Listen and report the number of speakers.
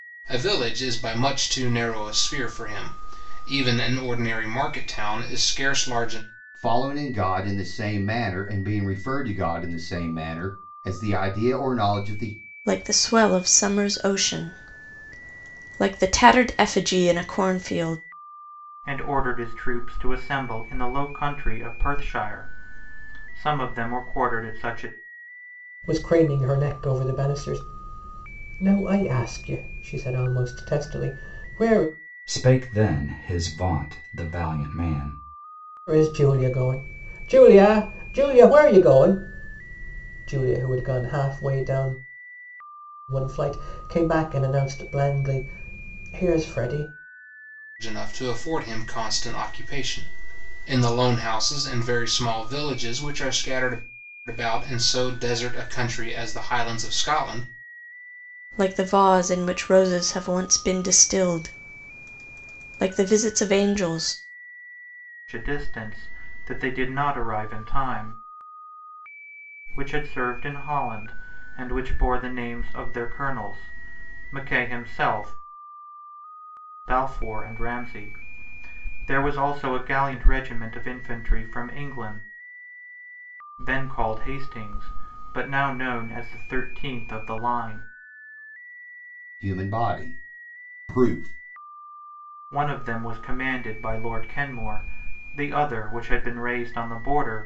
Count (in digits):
6